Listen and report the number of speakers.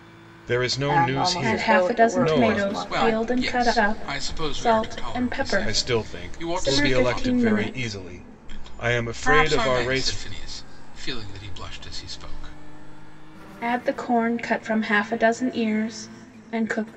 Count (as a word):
four